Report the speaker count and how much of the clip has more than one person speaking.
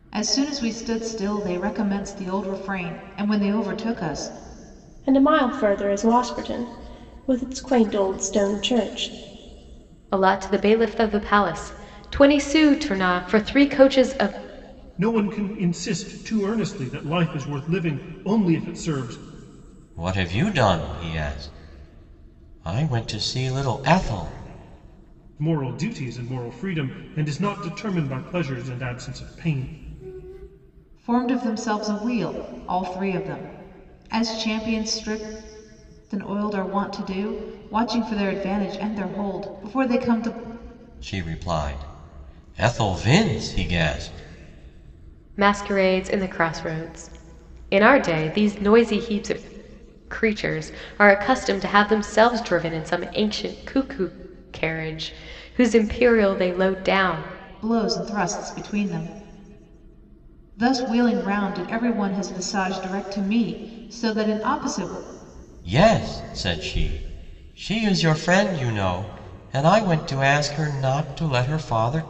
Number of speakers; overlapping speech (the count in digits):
5, no overlap